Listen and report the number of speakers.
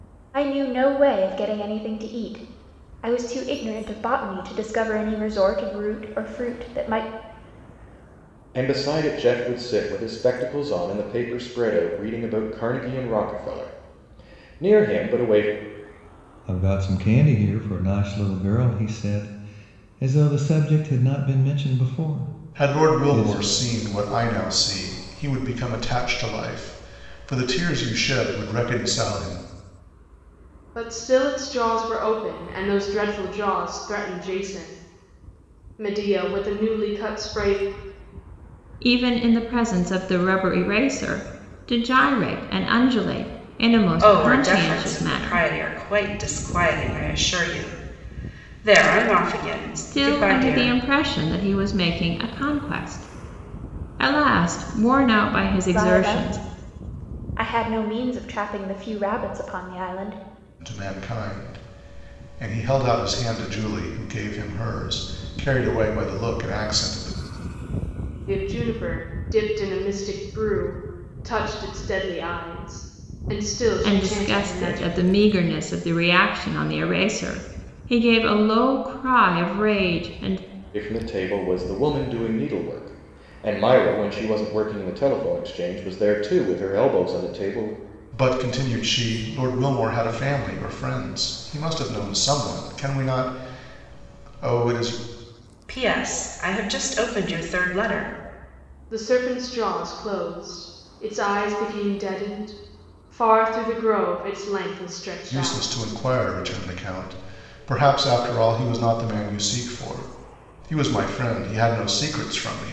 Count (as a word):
seven